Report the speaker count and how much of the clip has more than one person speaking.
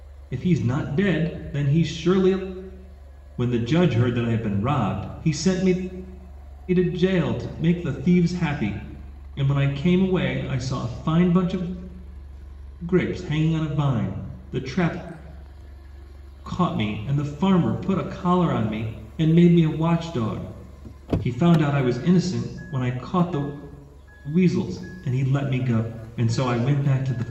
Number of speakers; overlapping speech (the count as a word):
one, no overlap